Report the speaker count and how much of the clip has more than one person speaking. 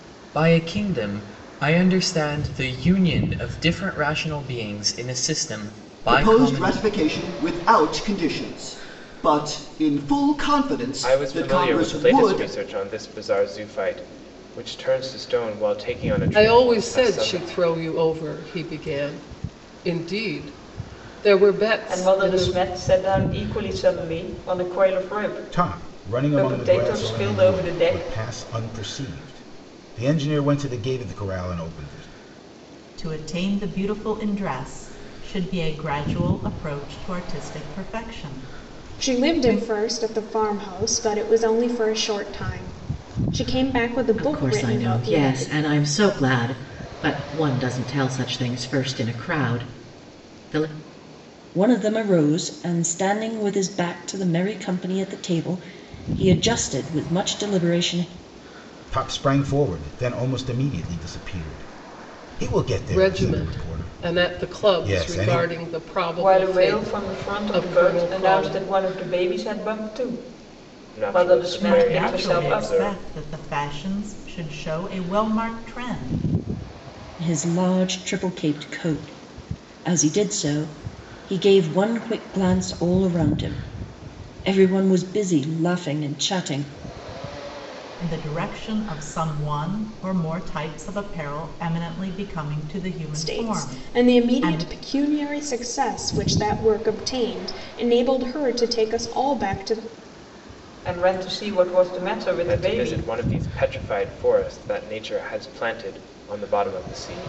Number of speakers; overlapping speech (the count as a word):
ten, about 17%